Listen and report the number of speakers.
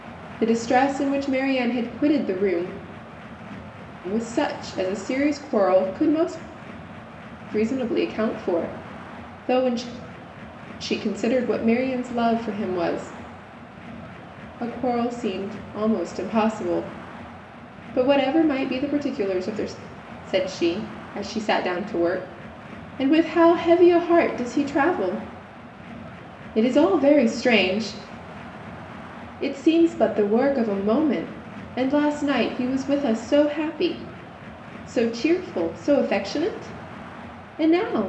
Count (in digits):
1